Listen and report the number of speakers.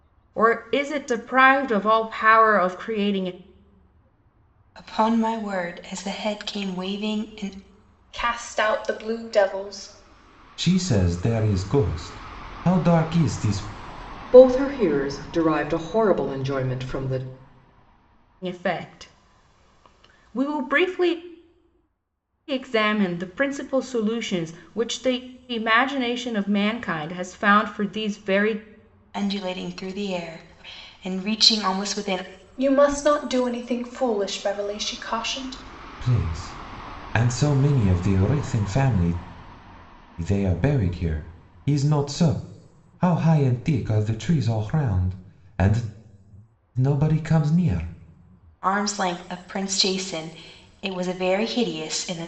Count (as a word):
five